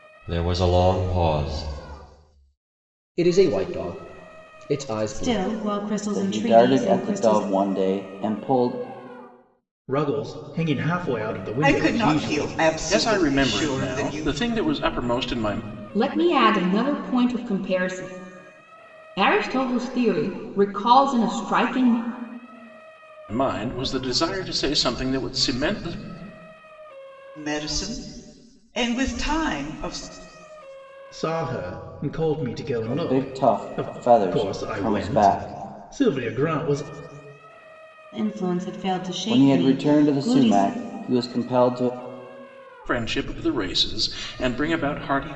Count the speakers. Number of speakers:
eight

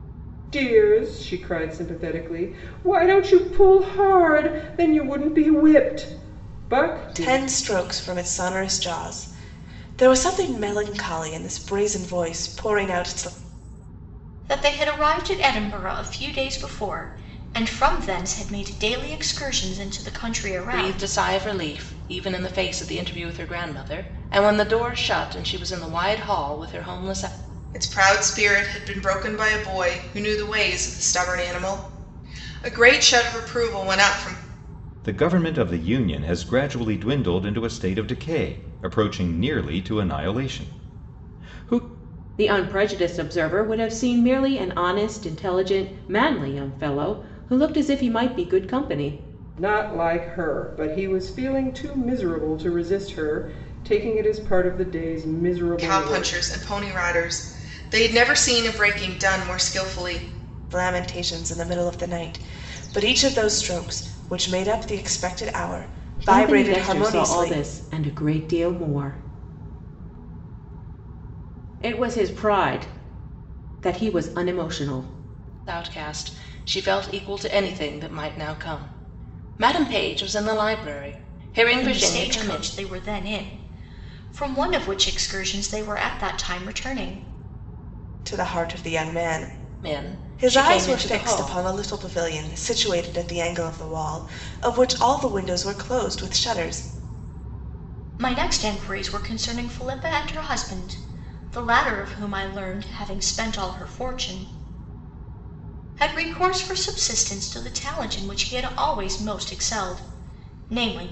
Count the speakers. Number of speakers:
seven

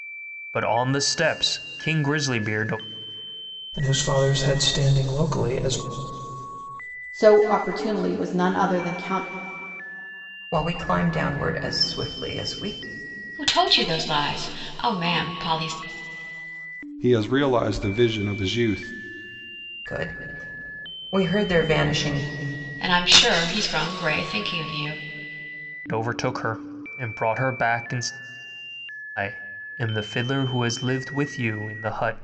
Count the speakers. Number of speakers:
six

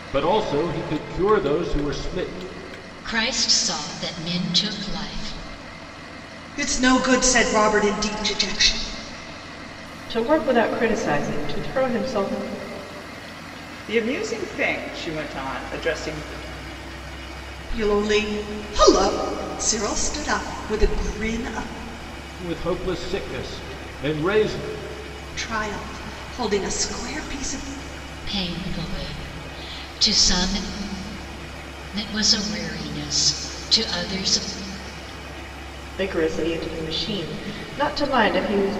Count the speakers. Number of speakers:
five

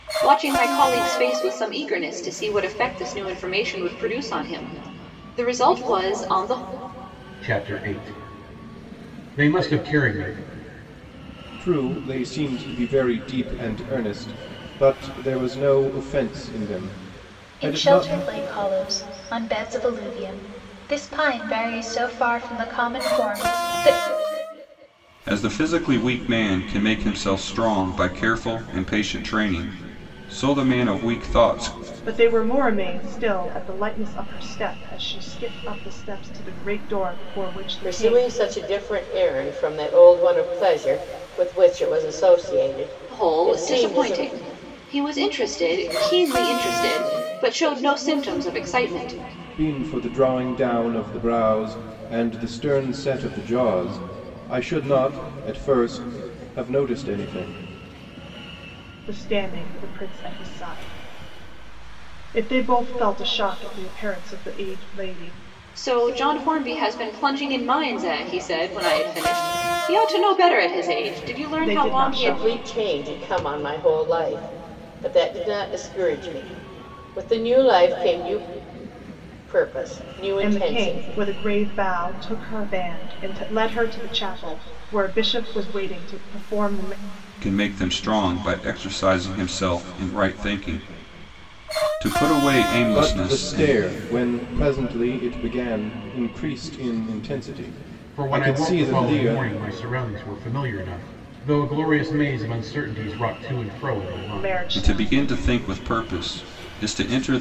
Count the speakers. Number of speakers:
seven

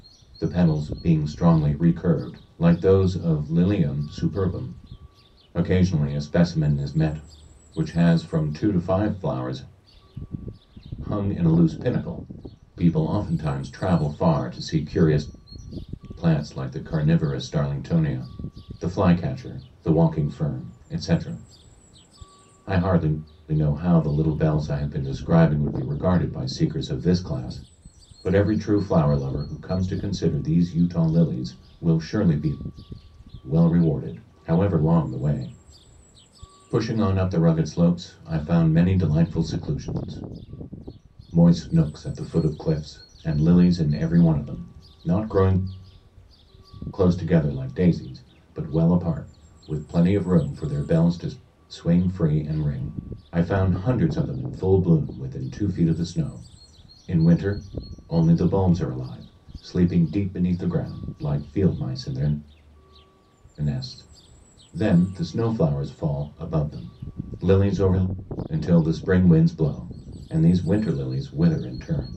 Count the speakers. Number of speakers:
one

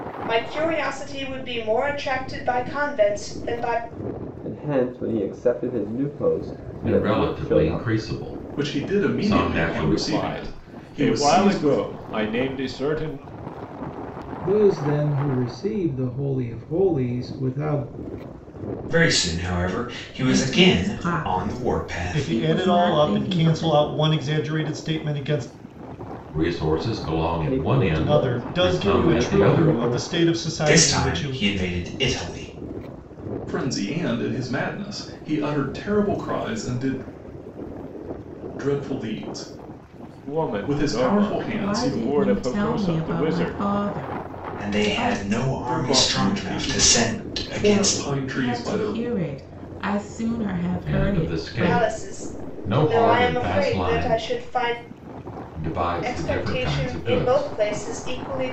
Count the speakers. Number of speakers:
nine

